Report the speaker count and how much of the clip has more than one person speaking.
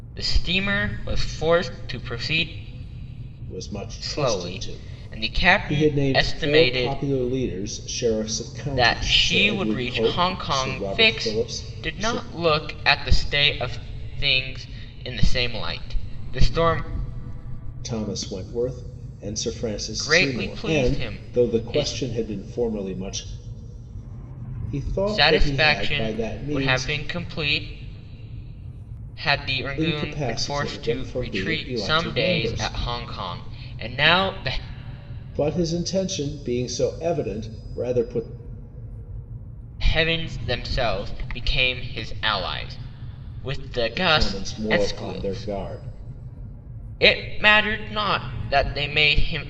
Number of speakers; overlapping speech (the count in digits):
2, about 31%